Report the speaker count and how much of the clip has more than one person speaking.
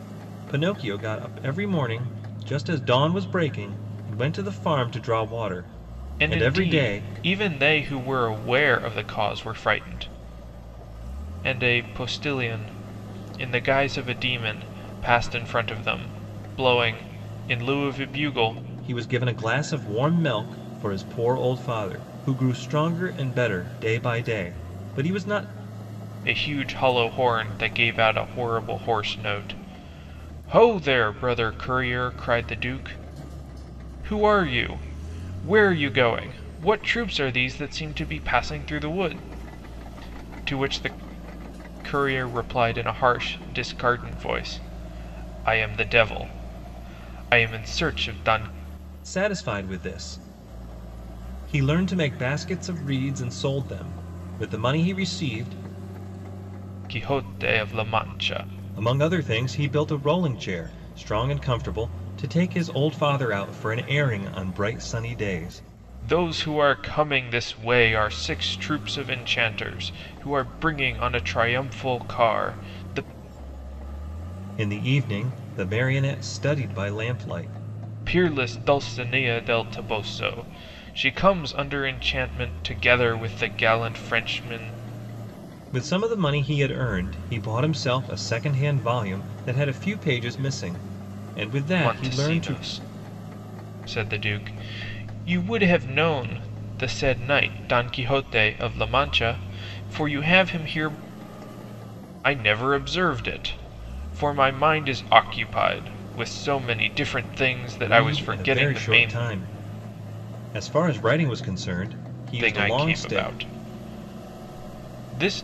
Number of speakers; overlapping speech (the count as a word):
two, about 4%